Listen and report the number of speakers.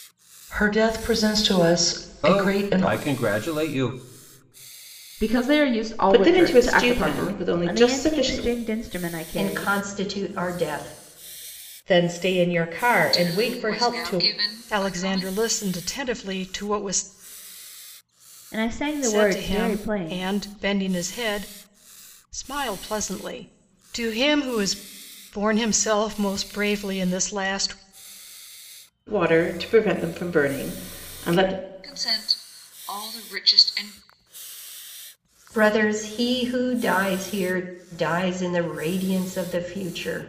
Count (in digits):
9